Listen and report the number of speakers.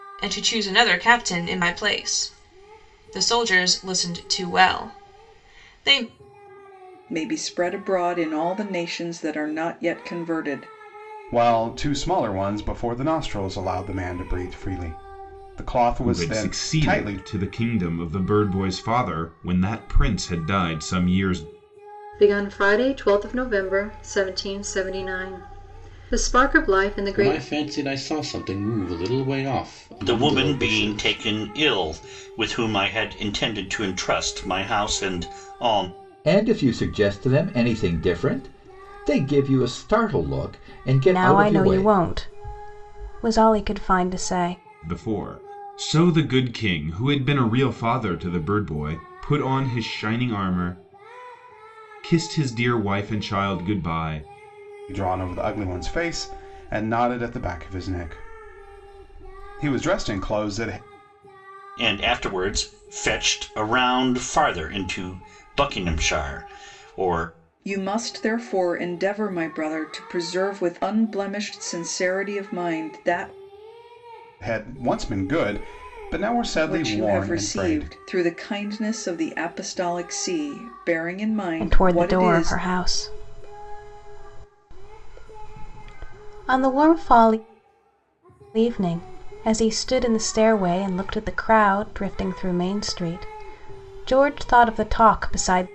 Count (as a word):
nine